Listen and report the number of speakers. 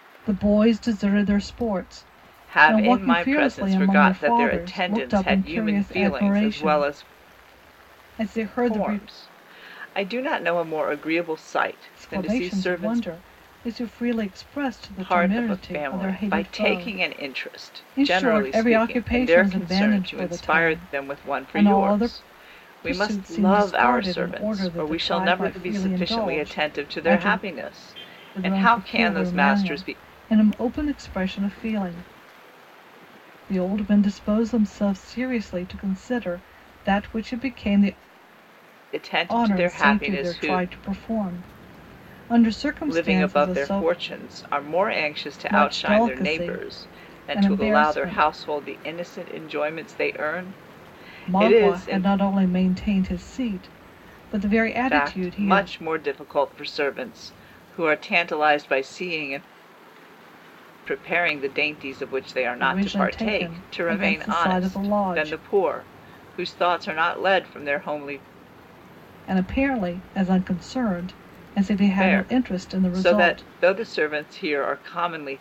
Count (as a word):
two